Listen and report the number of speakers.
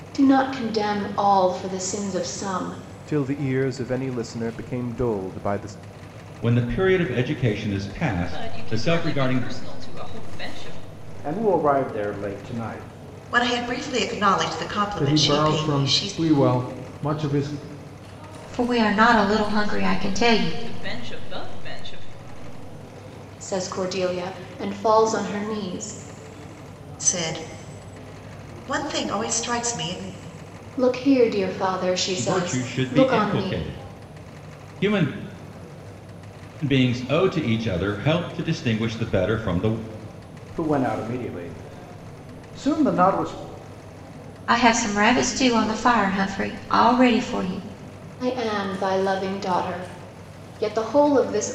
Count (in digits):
8